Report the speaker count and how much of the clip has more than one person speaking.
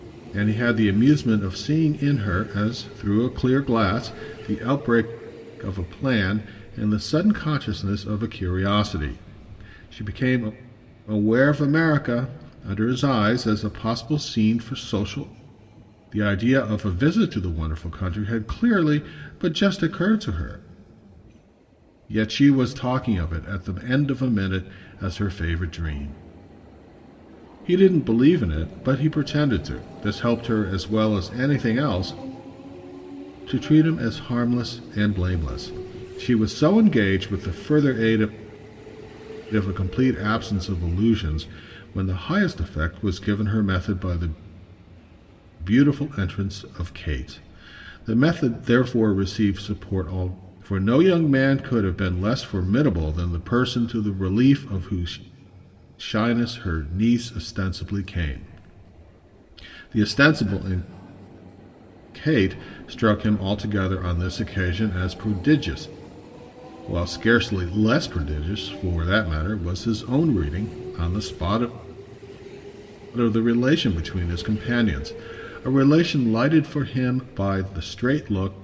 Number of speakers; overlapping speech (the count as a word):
one, no overlap